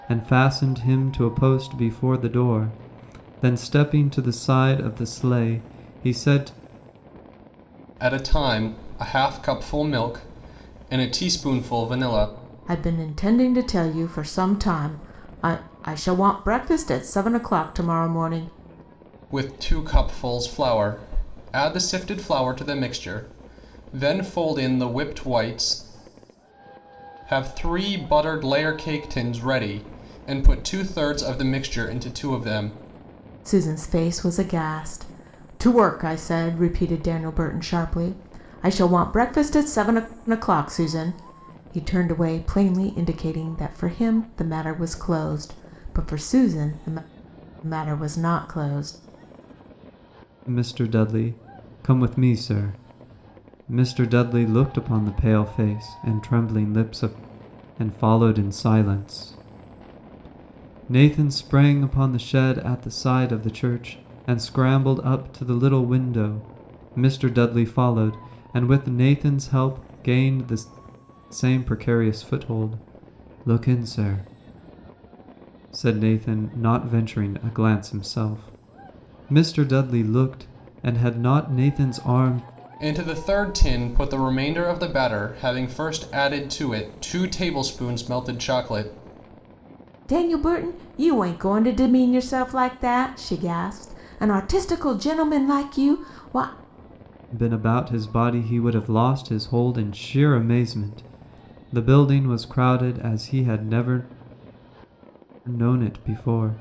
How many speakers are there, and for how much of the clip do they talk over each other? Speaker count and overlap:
three, no overlap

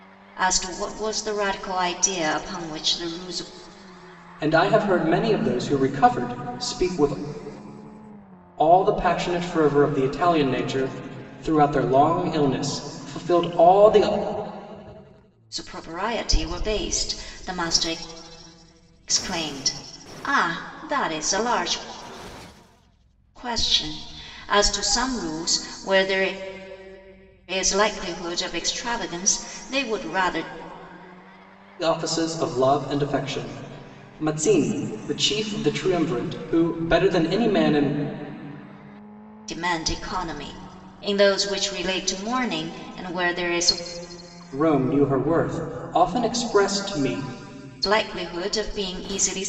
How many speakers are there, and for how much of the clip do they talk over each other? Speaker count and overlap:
two, no overlap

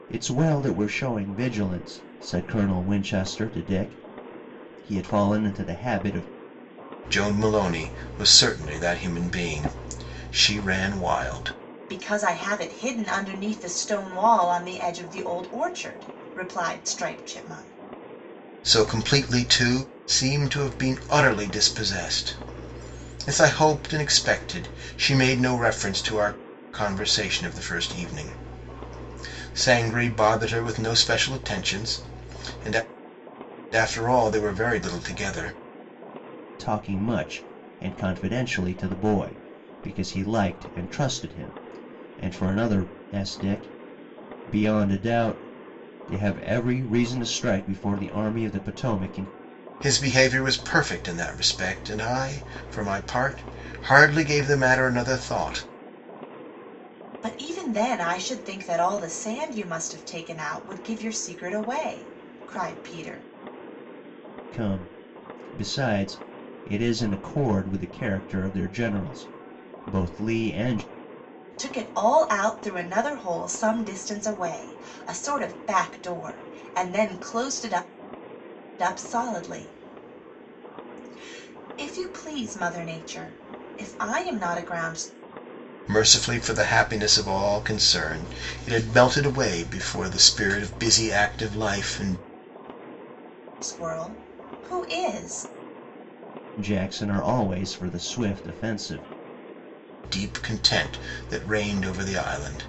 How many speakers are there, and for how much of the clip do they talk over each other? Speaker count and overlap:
three, no overlap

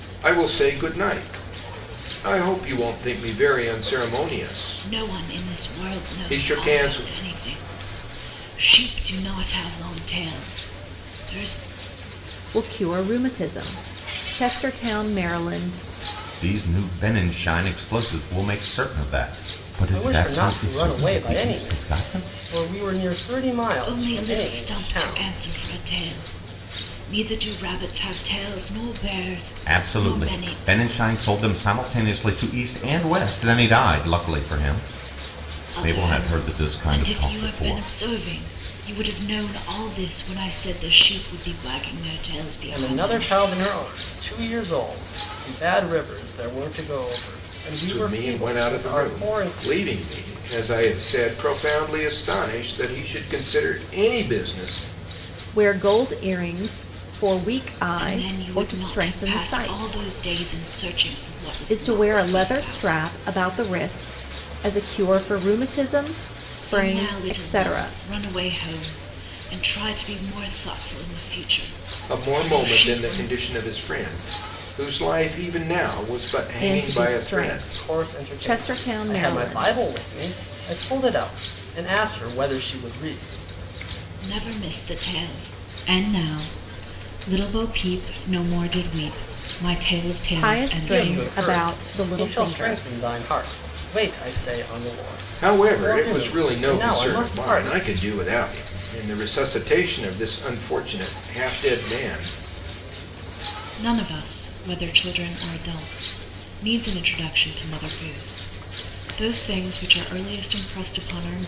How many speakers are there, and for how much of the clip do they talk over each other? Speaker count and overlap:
five, about 23%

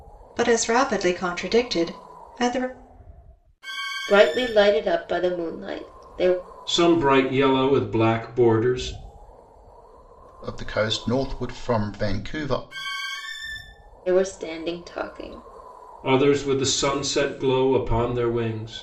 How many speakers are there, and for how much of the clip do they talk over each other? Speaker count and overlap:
four, no overlap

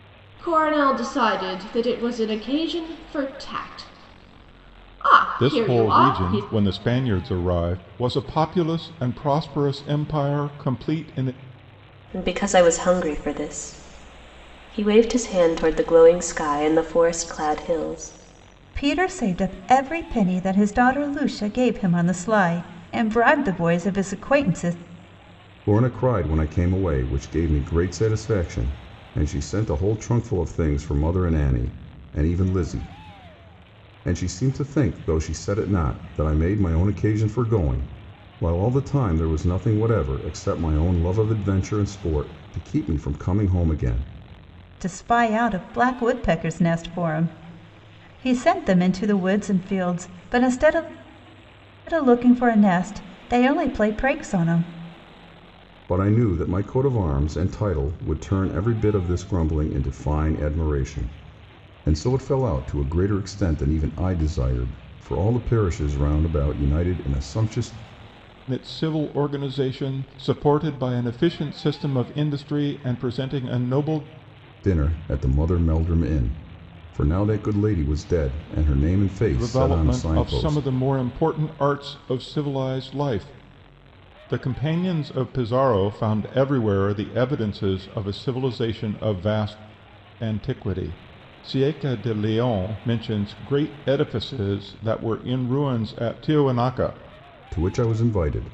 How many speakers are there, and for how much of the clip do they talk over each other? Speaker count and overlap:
five, about 3%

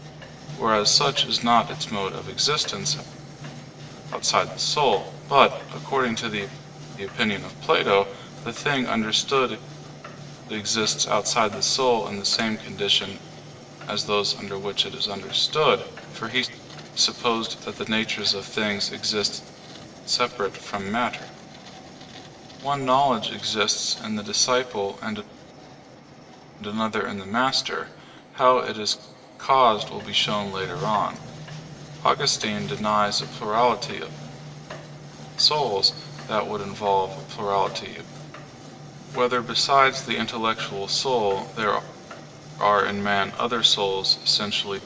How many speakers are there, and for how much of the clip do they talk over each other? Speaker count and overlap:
one, no overlap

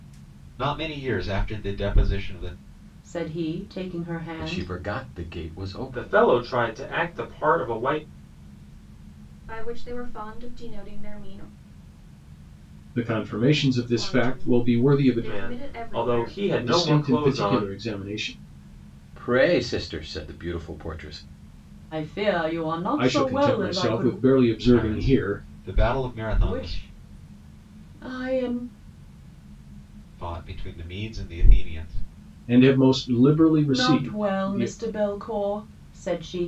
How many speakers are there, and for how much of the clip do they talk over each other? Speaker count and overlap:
six, about 21%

